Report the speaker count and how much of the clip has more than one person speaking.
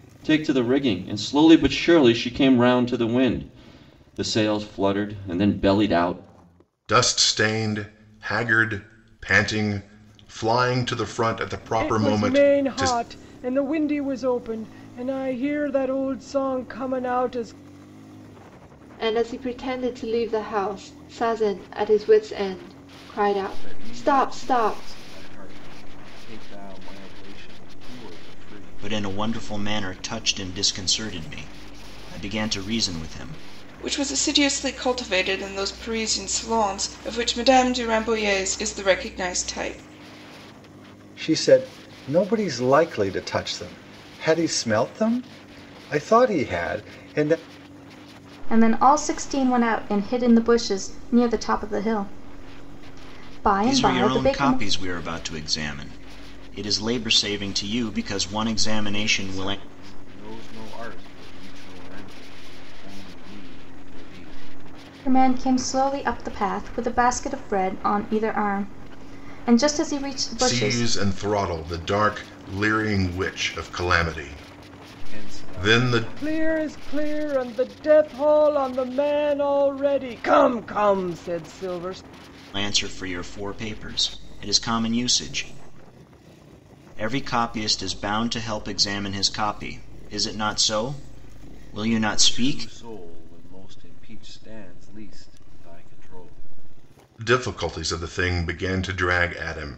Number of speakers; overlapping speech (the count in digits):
9, about 8%